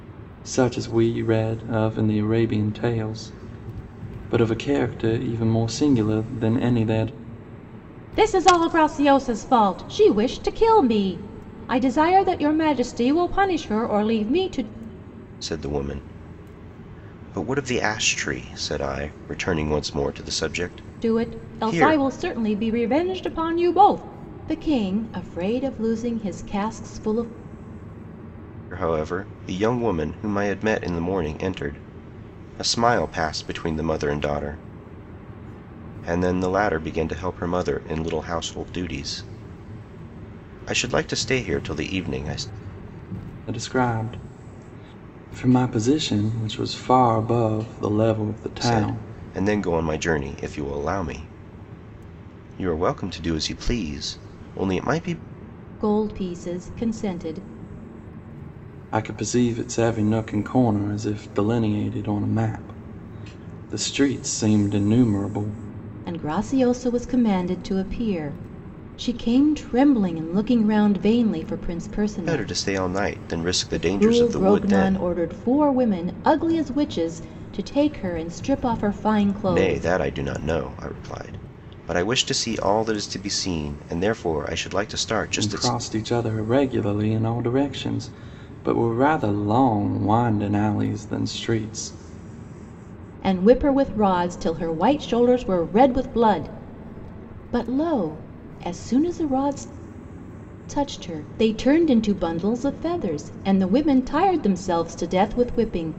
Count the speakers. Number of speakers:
three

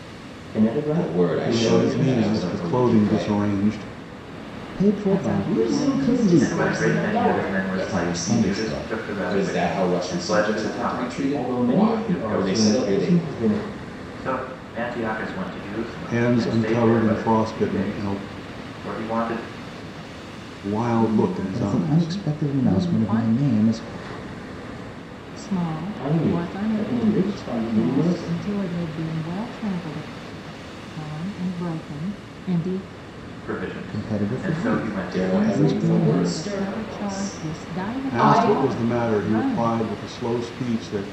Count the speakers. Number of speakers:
seven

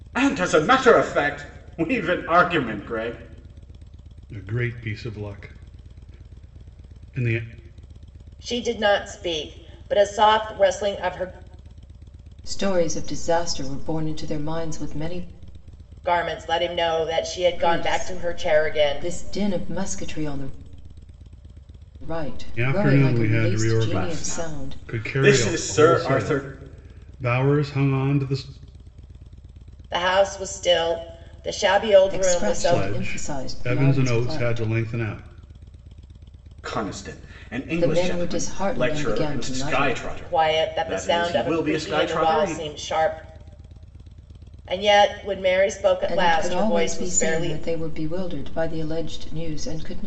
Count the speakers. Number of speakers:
four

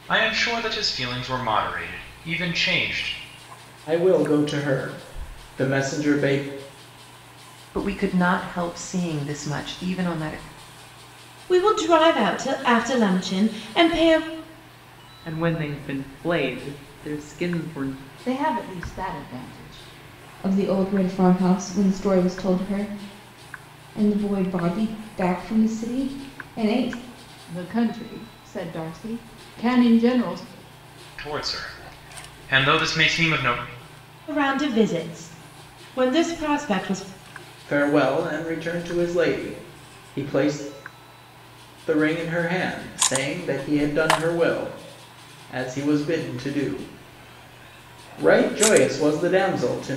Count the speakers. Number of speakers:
seven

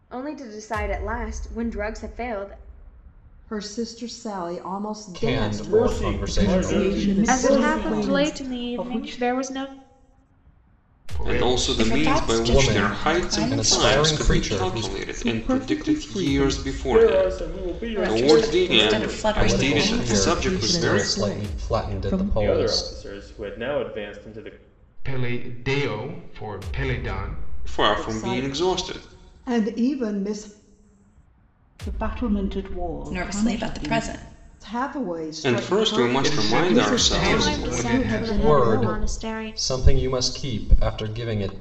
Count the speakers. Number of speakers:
ten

